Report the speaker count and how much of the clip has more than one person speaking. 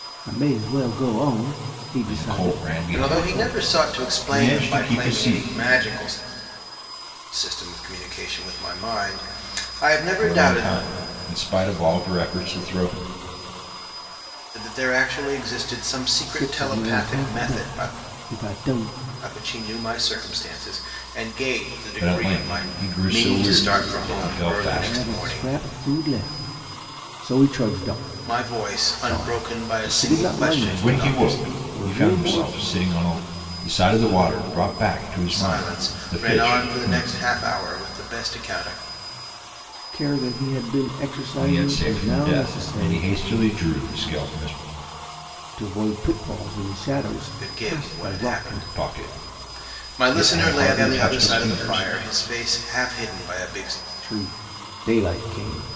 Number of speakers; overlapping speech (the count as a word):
three, about 37%